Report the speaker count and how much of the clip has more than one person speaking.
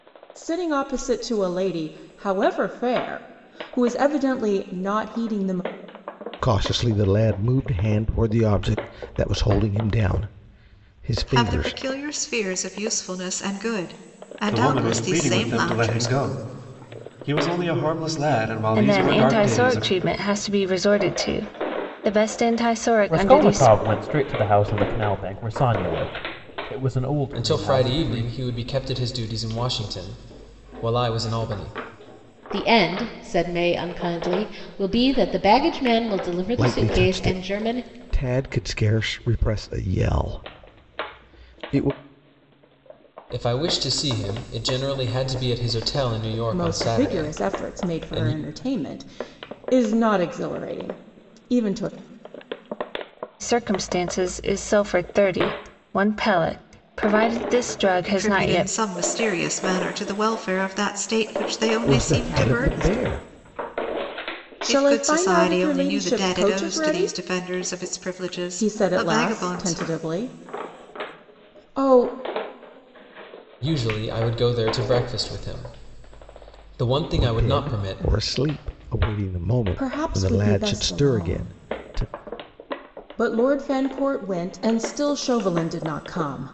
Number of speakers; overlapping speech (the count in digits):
8, about 20%